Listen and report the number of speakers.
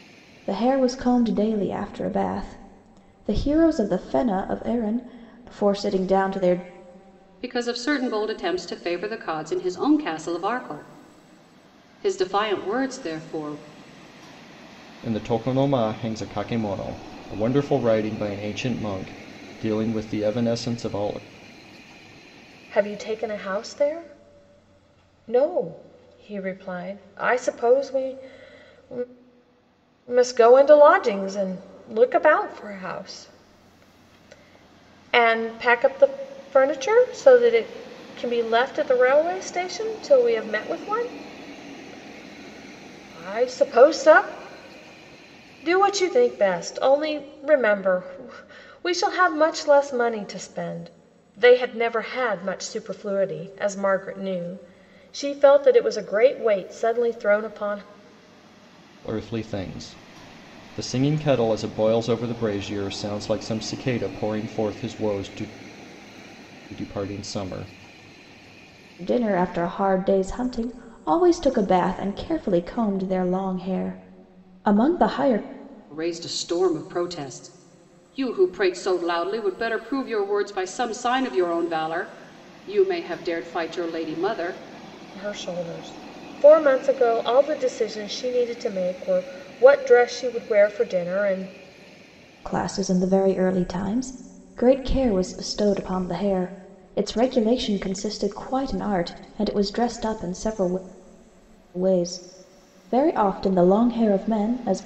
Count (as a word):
four